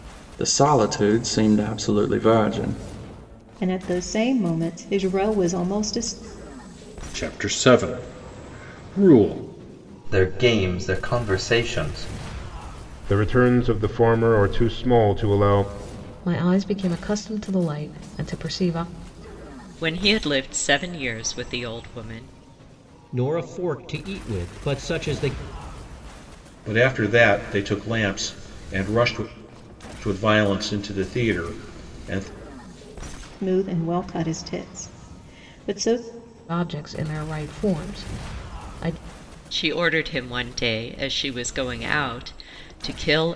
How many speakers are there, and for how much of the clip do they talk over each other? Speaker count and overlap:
nine, no overlap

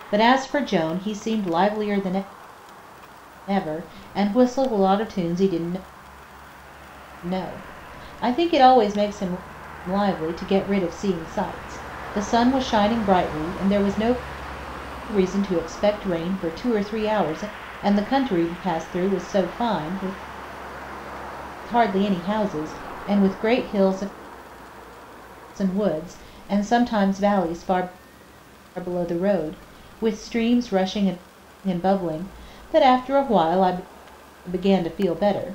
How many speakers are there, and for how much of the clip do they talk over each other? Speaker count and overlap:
one, no overlap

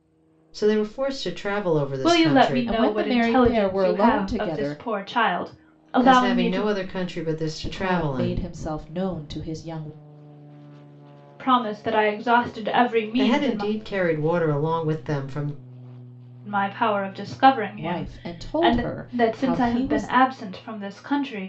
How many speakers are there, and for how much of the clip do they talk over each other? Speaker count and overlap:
three, about 33%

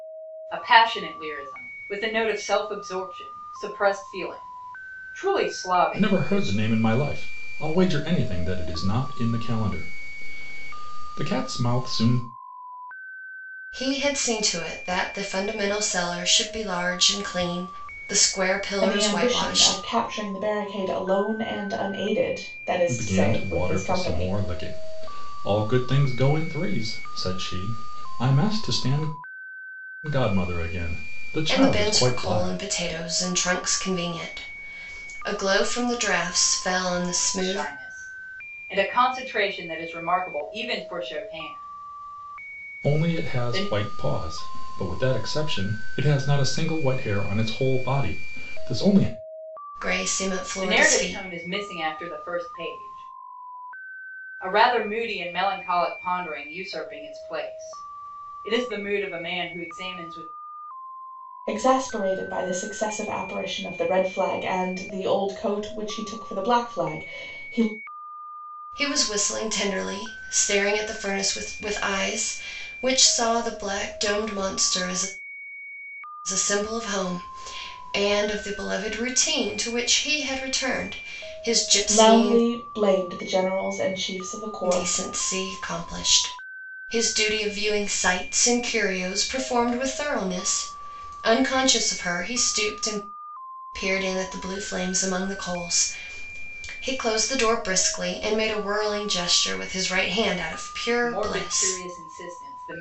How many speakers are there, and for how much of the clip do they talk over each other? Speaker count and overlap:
four, about 8%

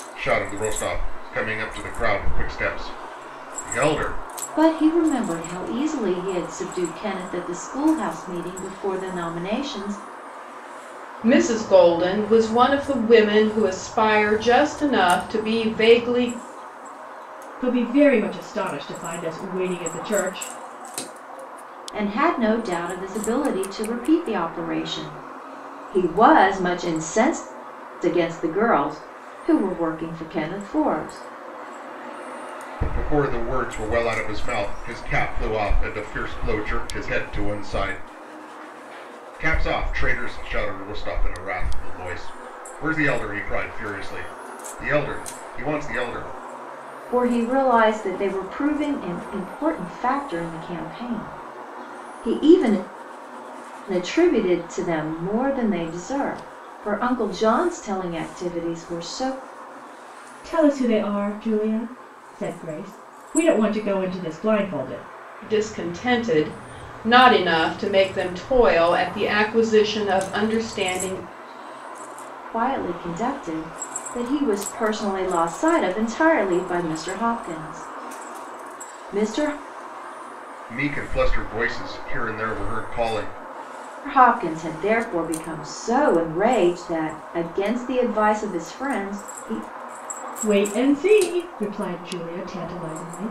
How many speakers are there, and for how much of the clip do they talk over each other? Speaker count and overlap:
four, no overlap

